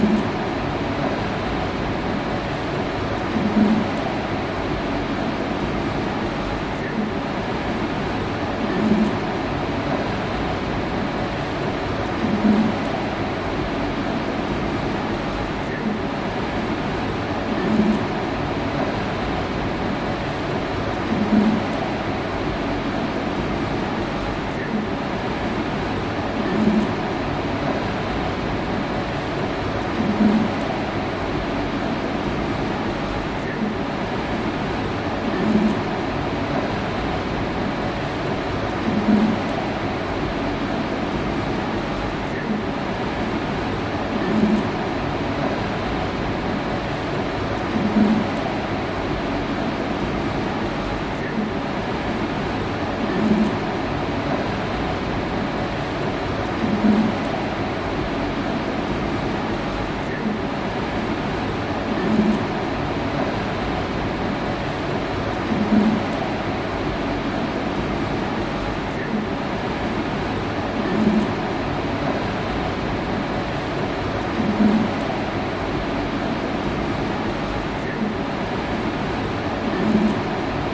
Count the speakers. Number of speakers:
0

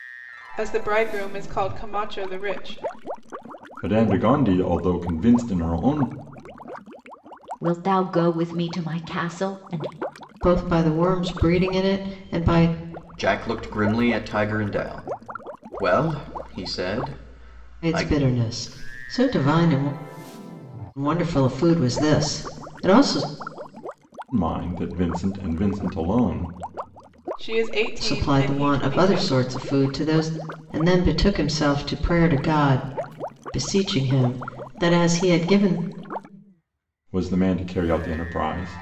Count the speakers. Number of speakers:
5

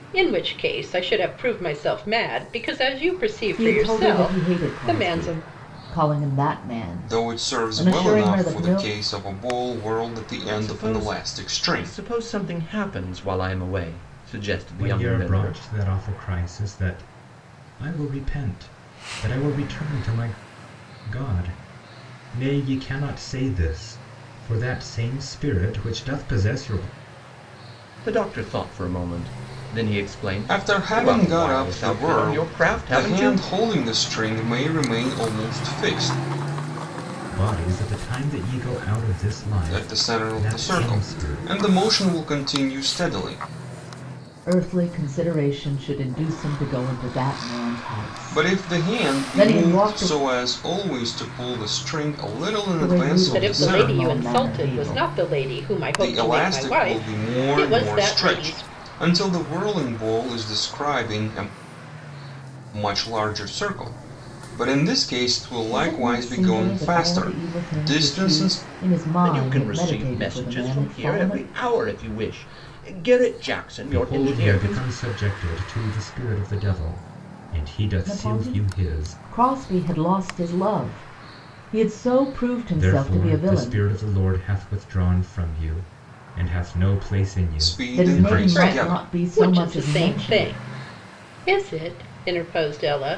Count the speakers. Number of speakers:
5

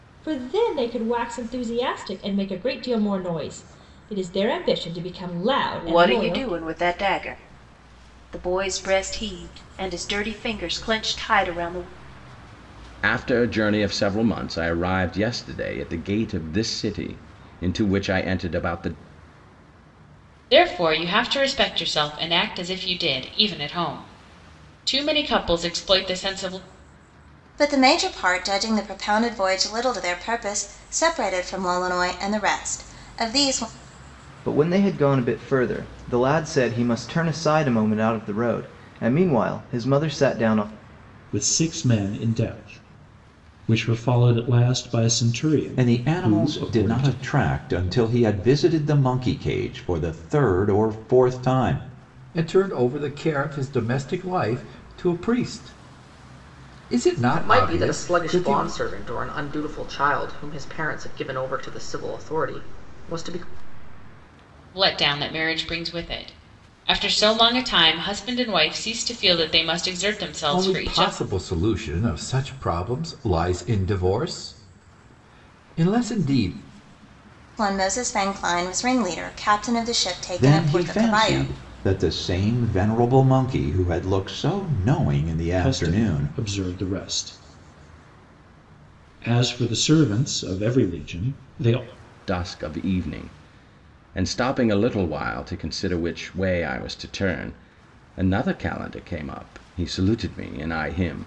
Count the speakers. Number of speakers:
10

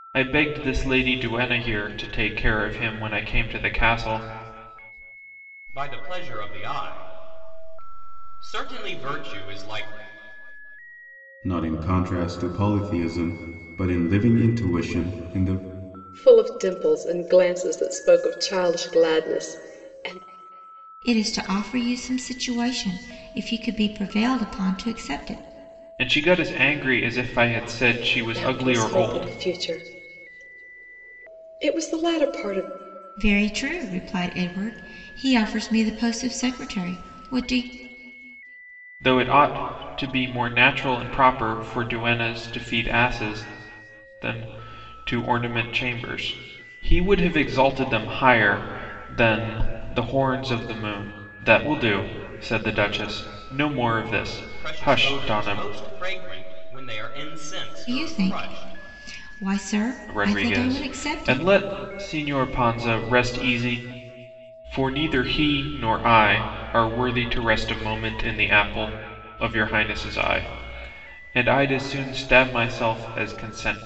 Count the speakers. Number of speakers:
5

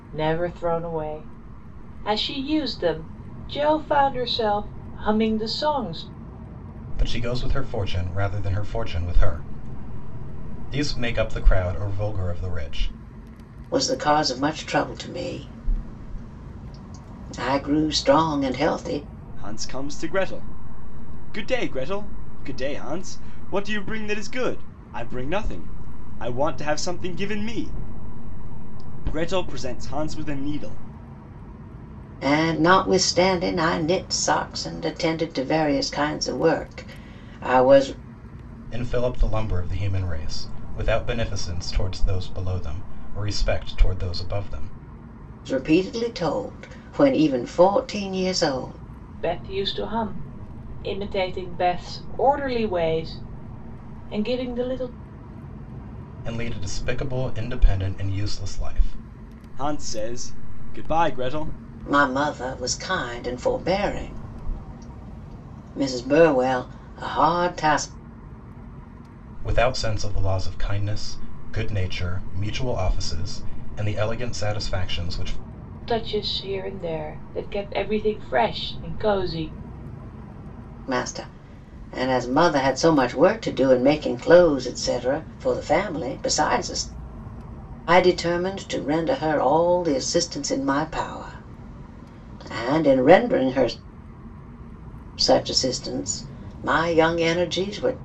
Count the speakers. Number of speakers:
4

